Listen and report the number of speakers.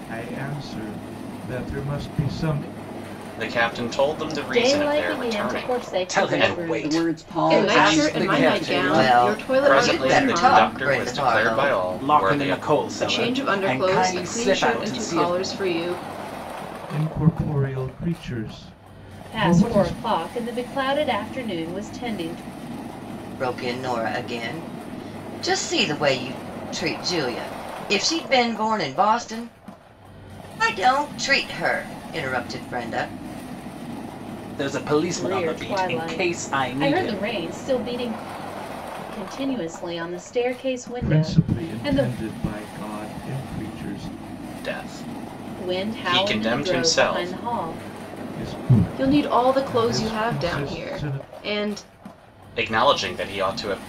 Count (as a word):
seven